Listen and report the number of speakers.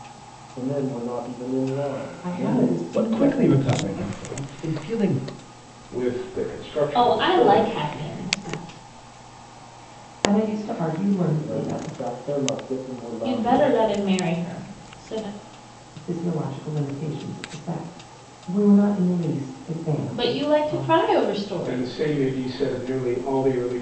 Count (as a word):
six